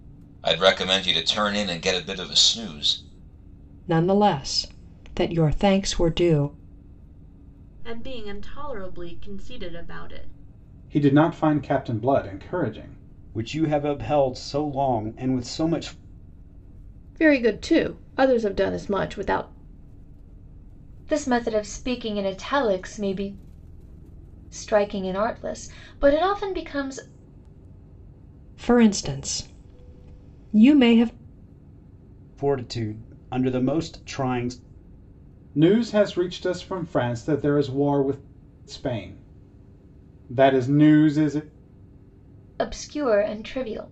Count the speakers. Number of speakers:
7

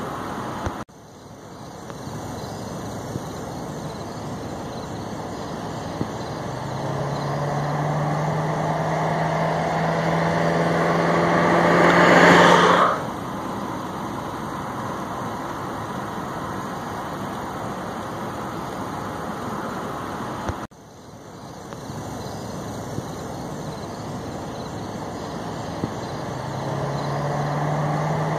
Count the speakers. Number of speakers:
0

